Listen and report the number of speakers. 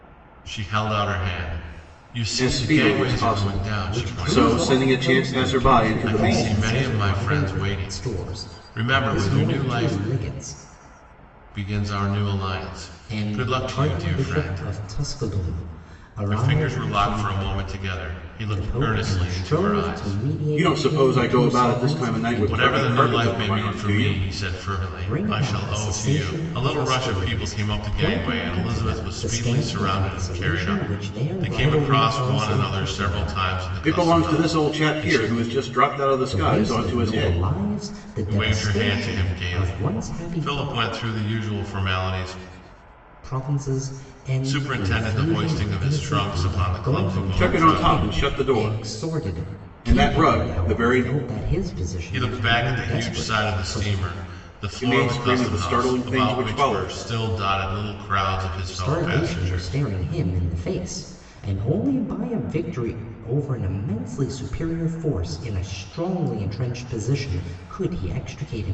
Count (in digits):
3